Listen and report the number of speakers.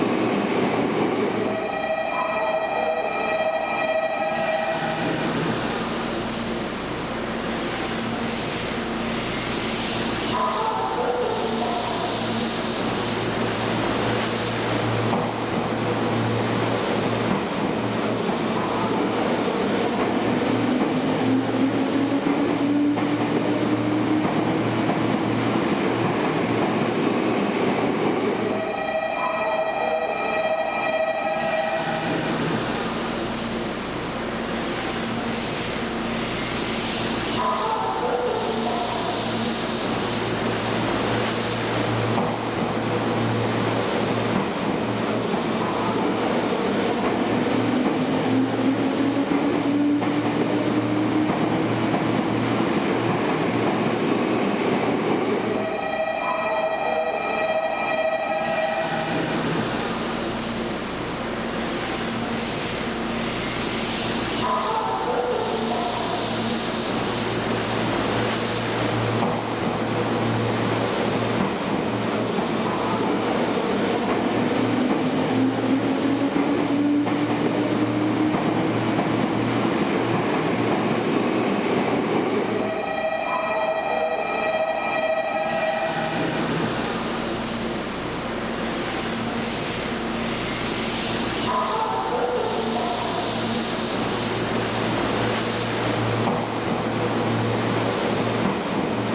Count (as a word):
zero